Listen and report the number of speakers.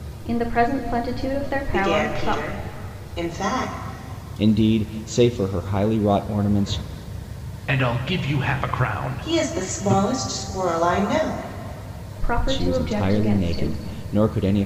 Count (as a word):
four